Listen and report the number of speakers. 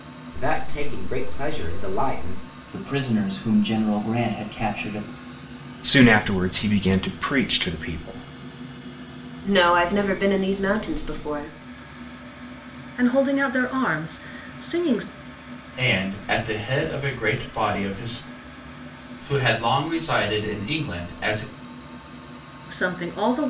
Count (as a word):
six